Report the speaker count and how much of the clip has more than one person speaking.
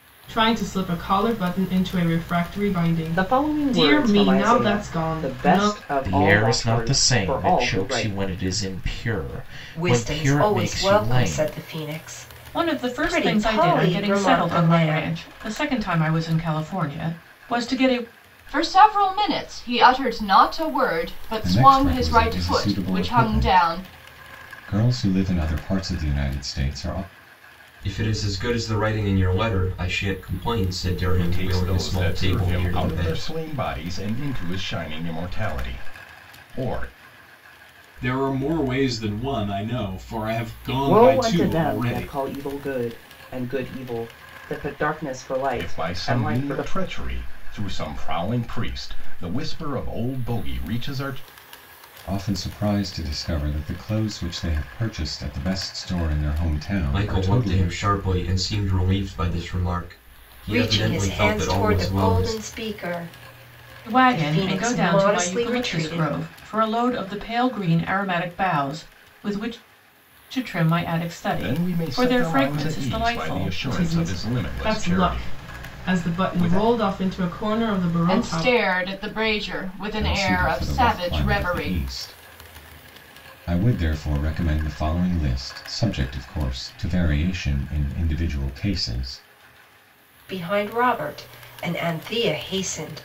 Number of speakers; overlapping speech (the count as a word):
ten, about 31%